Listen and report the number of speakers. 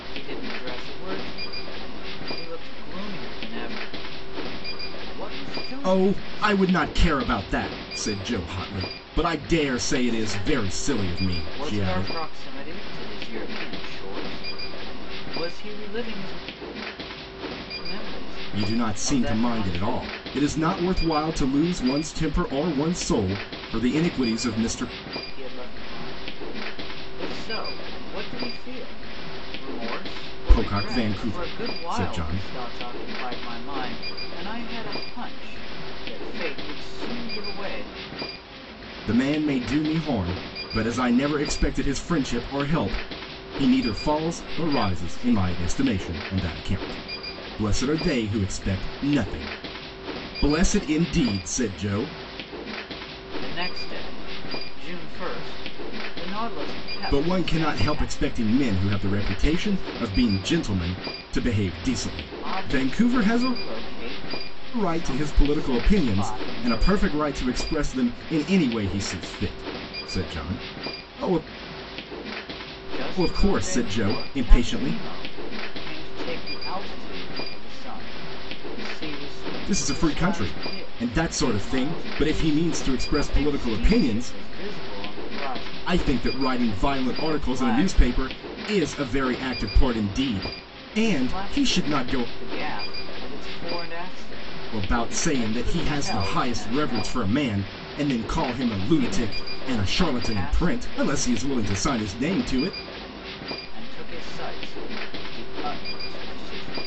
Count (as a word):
two